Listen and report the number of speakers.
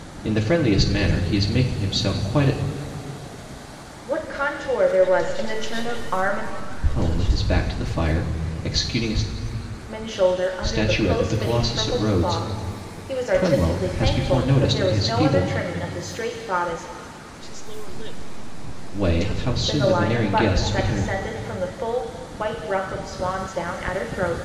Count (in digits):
3